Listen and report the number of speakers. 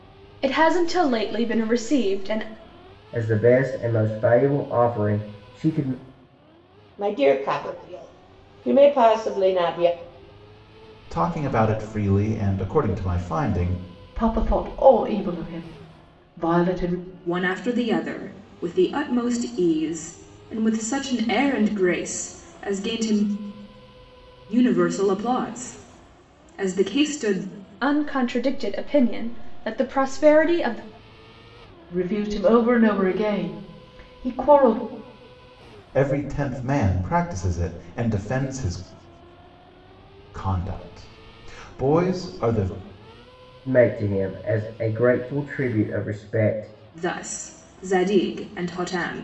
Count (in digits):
6